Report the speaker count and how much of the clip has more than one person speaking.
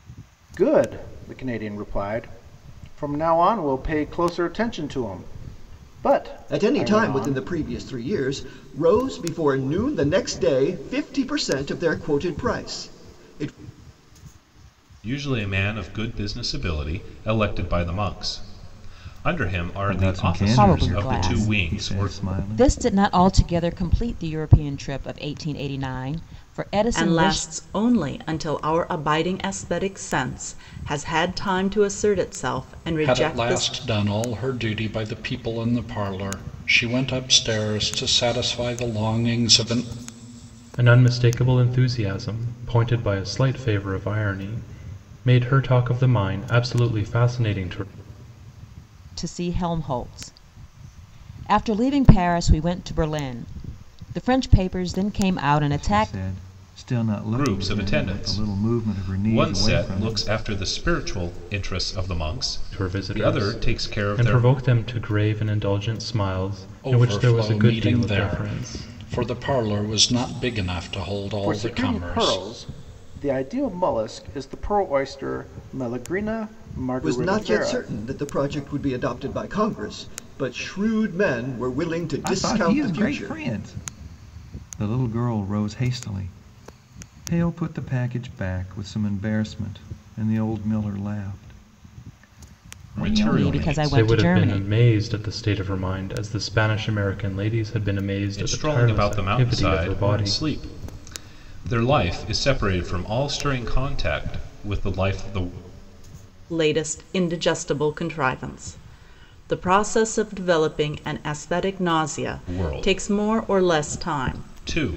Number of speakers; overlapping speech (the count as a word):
eight, about 19%